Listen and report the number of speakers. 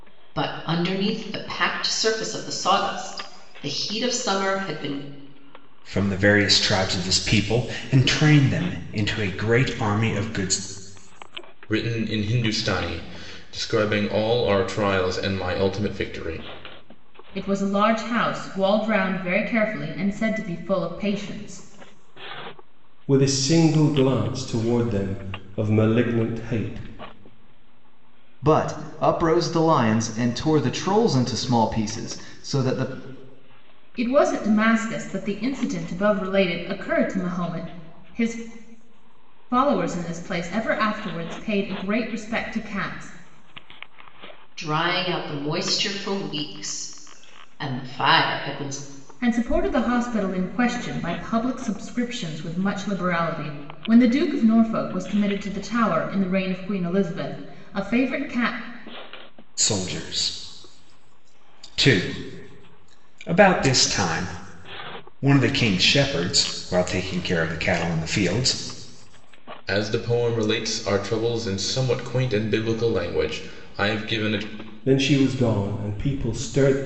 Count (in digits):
6